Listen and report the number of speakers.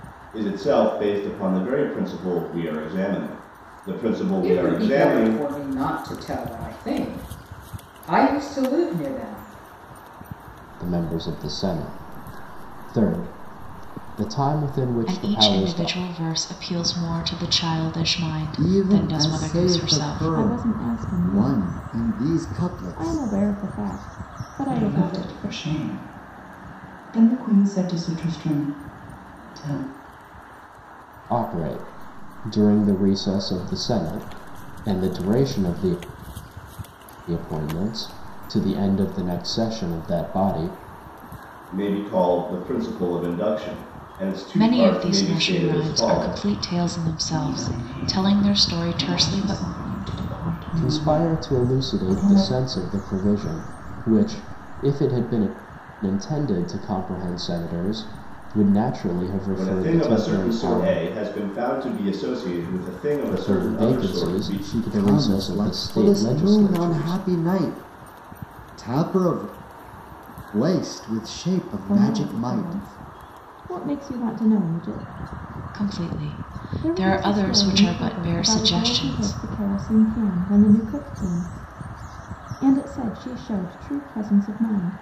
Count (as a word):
seven